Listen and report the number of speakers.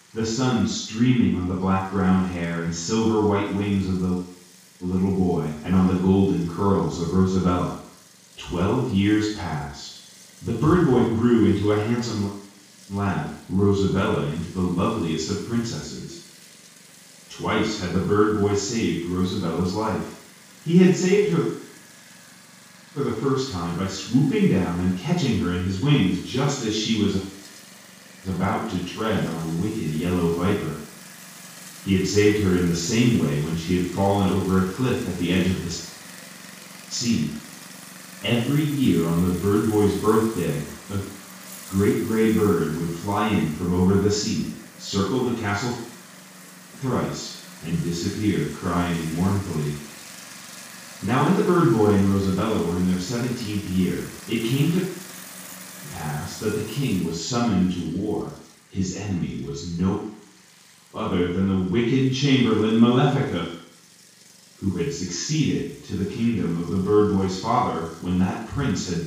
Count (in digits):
1